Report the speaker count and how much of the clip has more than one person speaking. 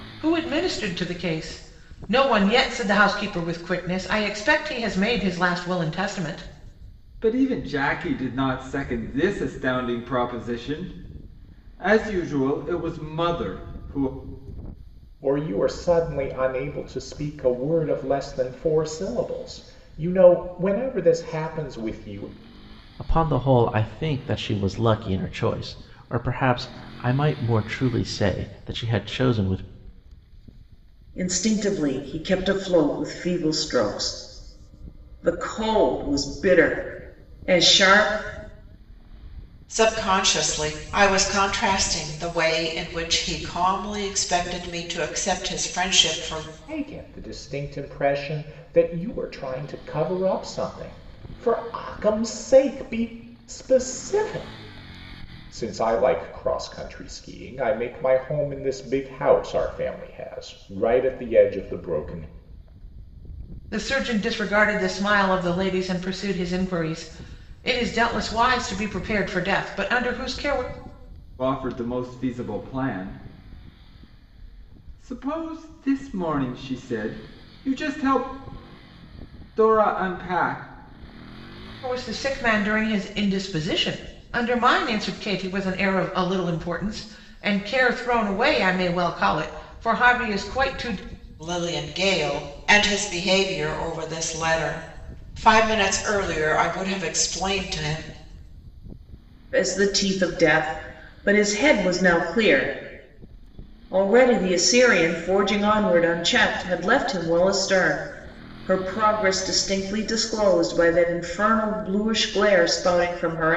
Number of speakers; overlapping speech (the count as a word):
six, no overlap